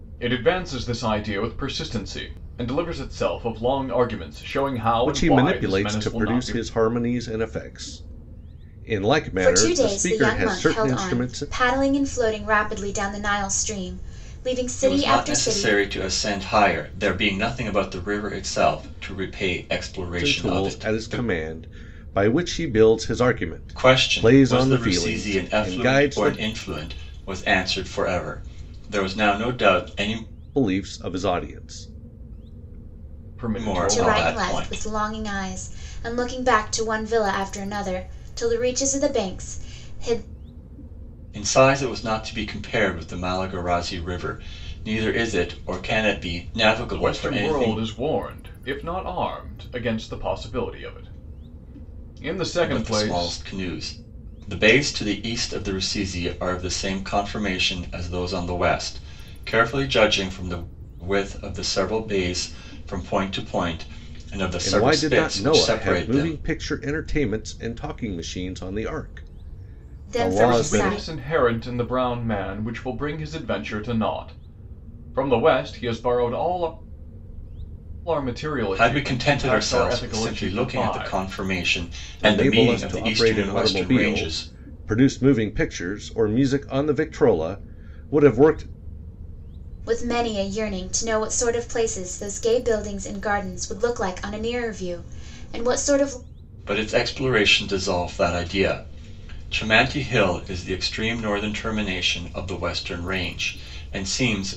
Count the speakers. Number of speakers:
four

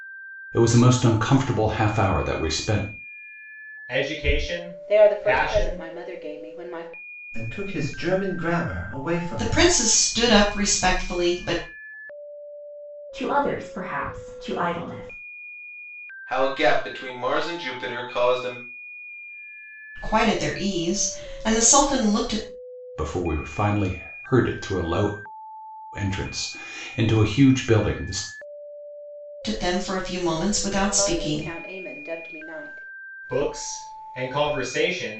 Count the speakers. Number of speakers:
seven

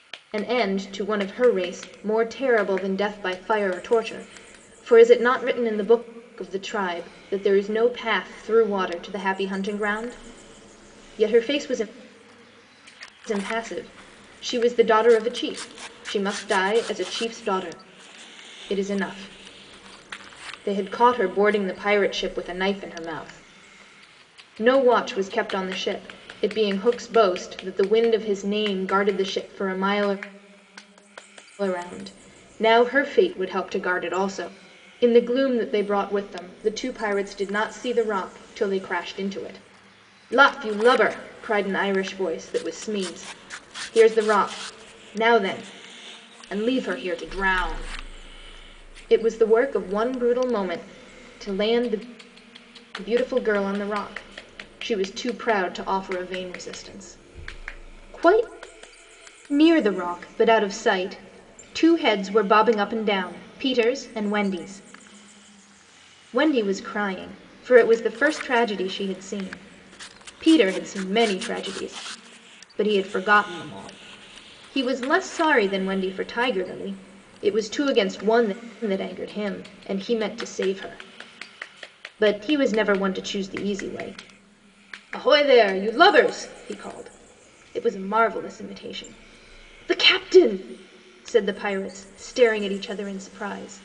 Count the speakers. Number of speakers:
one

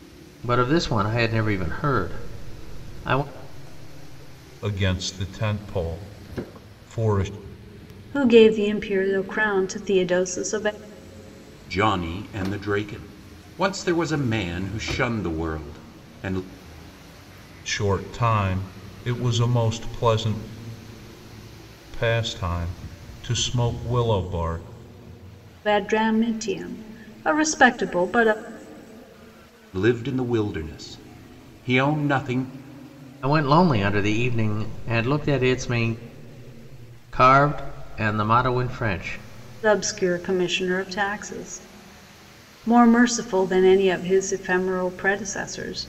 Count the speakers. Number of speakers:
four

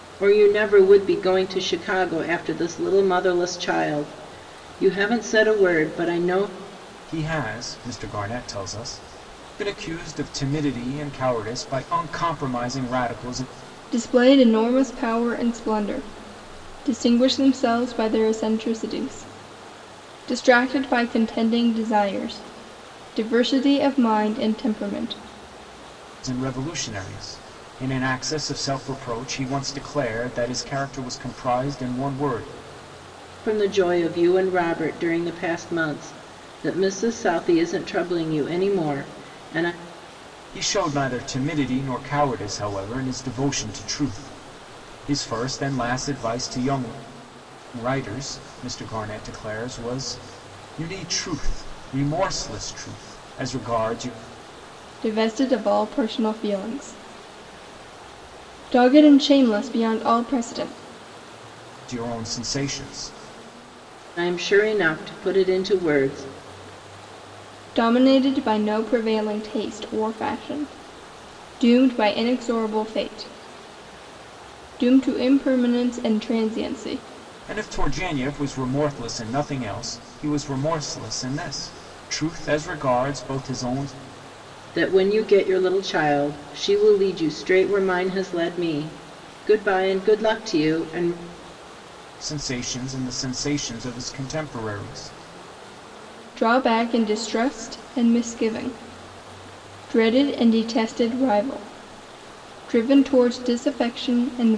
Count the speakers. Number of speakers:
three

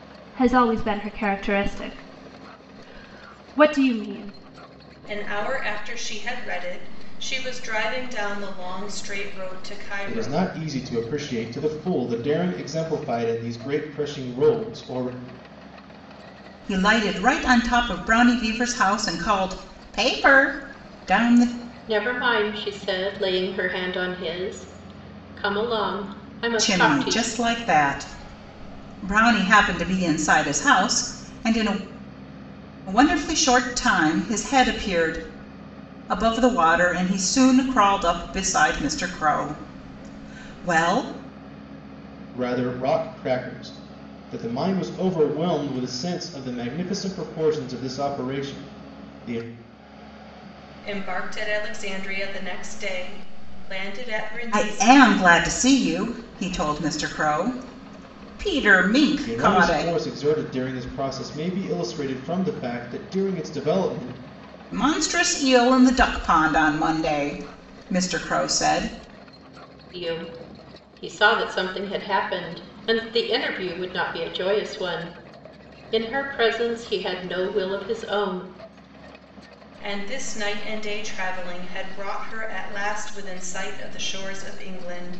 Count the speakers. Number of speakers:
five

